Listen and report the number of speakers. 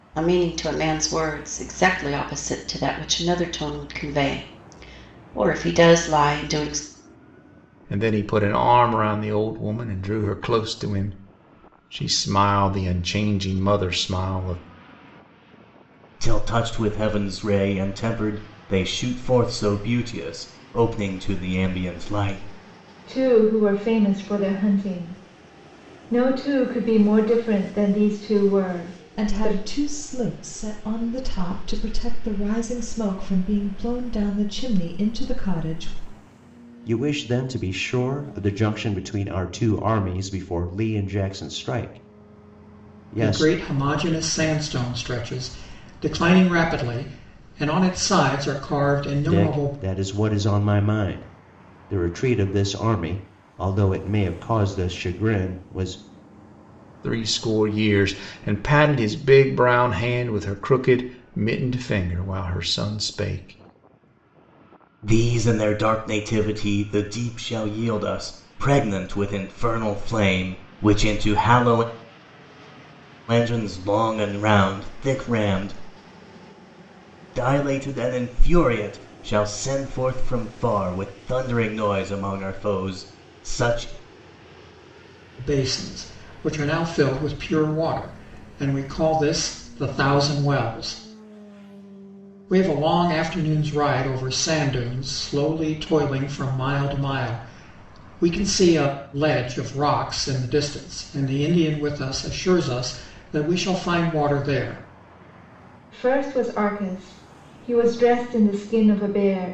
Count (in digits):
7